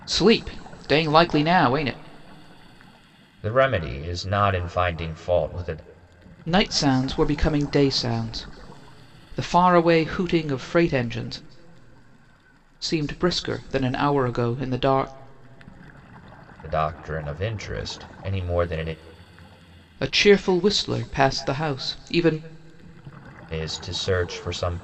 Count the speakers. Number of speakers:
two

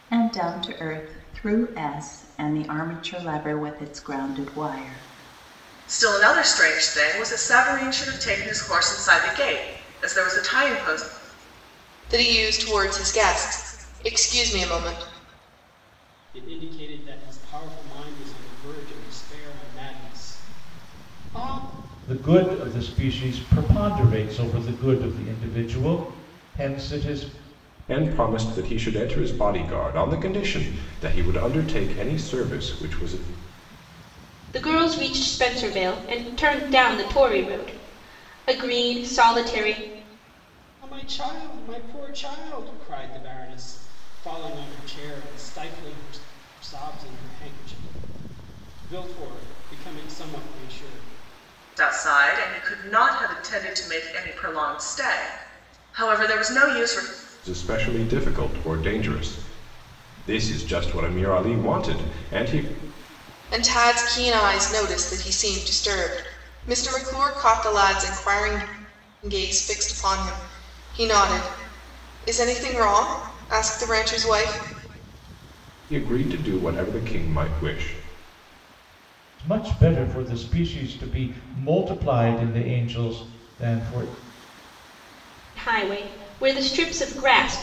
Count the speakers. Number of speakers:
seven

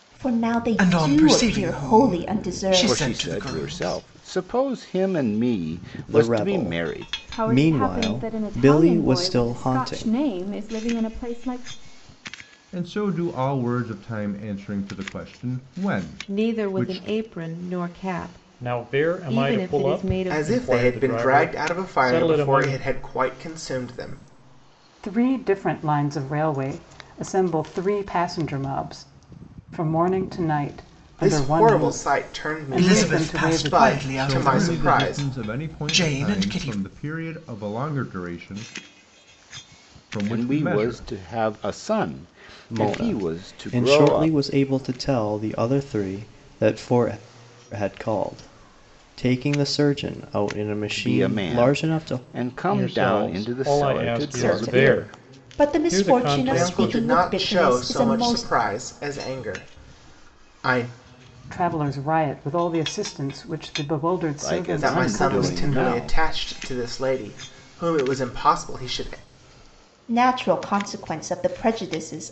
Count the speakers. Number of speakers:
ten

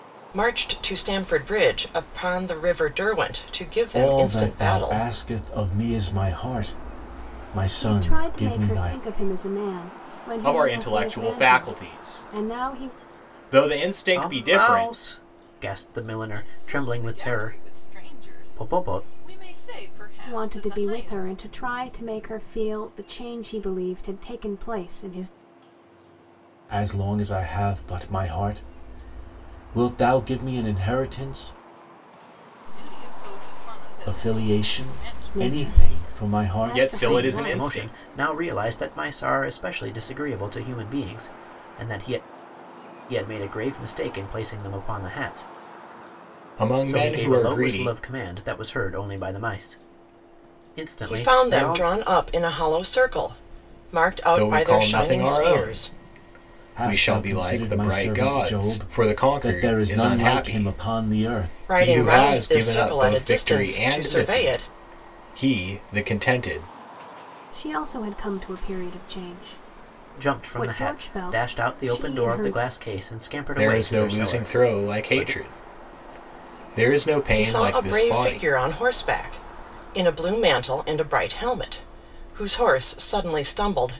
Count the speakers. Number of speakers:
six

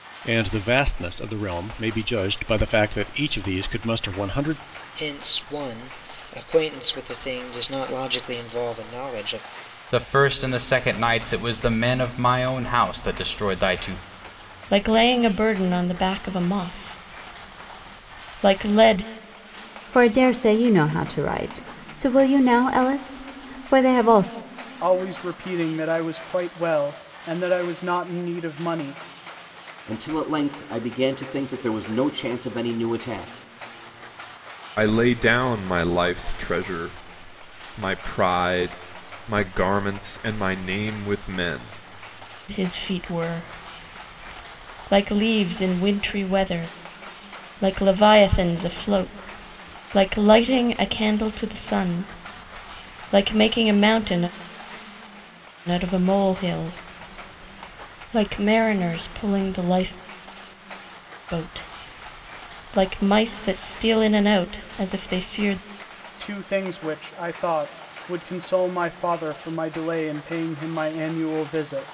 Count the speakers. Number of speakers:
eight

